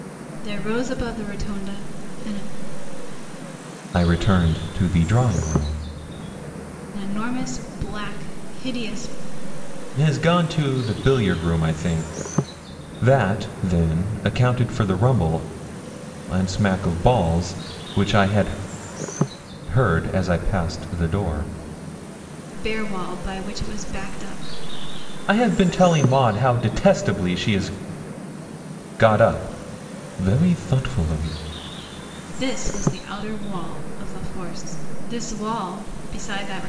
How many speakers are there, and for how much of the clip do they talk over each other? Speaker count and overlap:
two, no overlap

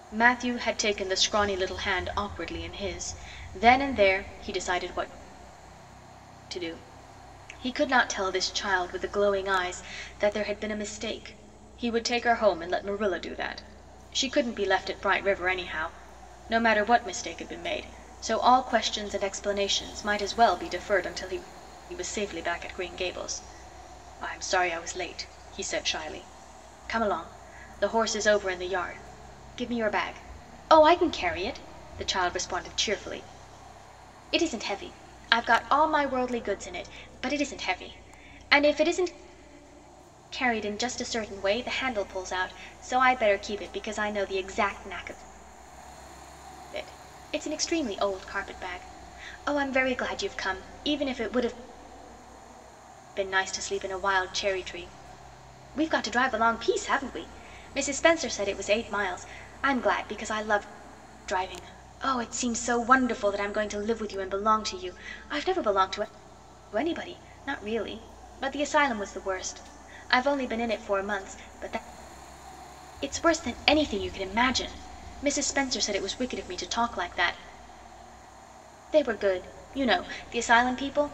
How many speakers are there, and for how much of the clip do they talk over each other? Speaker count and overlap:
one, no overlap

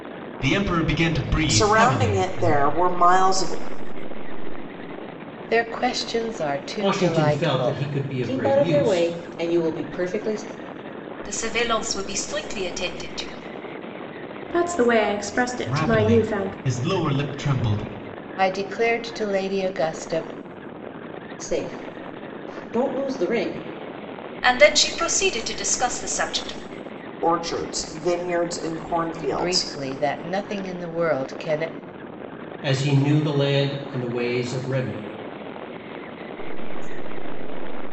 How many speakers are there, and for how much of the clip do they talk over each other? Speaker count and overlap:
eight, about 14%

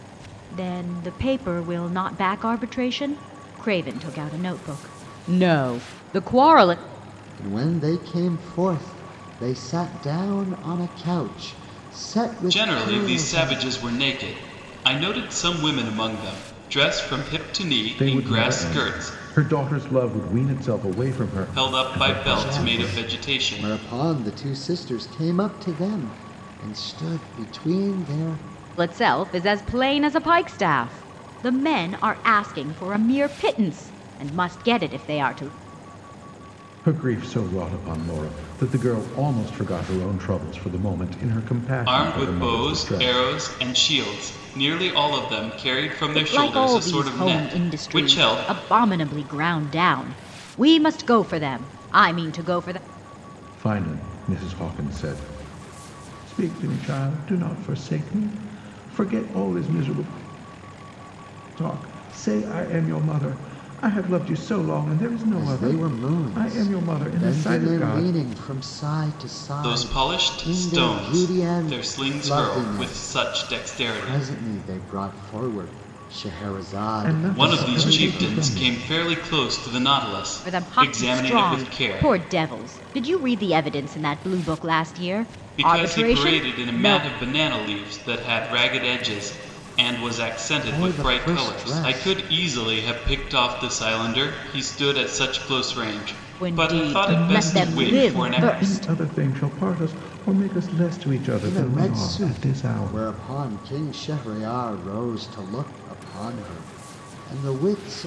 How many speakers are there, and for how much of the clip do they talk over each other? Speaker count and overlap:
four, about 24%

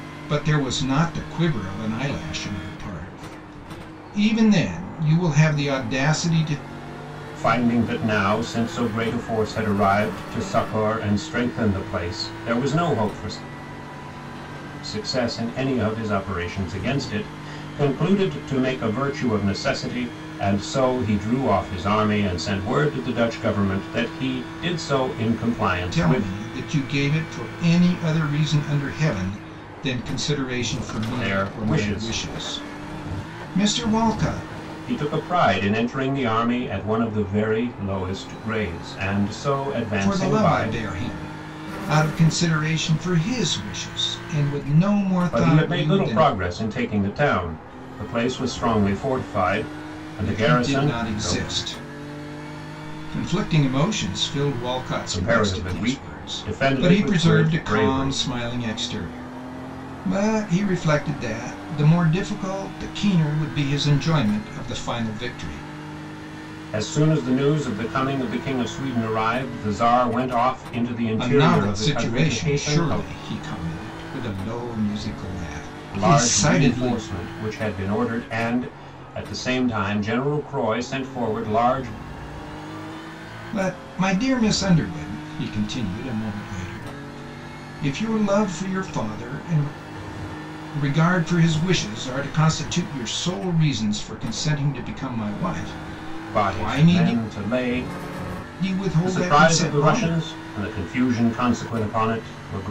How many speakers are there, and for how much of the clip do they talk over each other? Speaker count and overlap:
two, about 12%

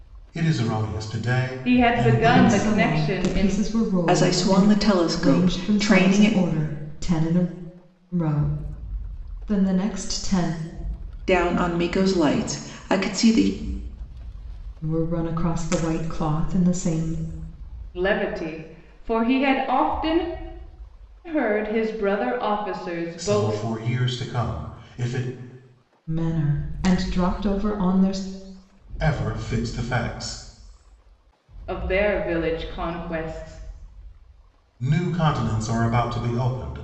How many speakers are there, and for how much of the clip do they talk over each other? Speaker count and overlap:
four, about 12%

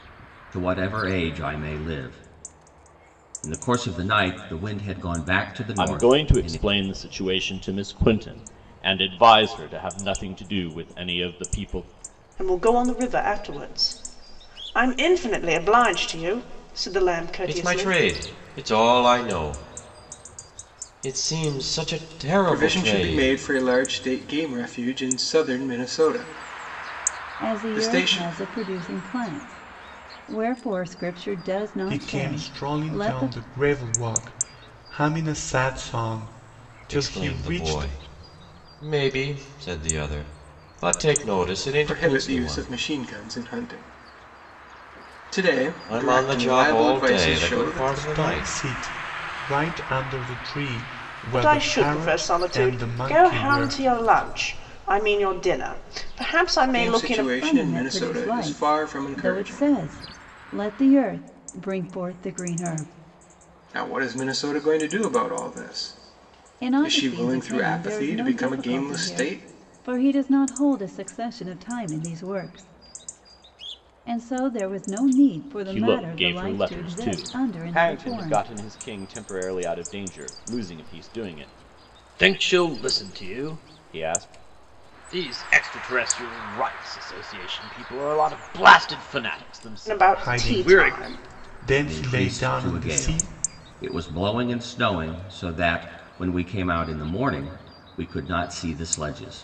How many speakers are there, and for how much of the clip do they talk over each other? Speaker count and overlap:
seven, about 24%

